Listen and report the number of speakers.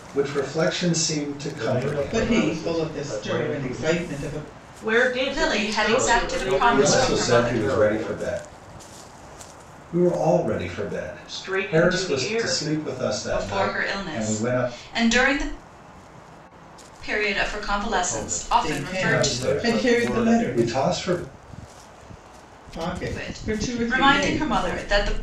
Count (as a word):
five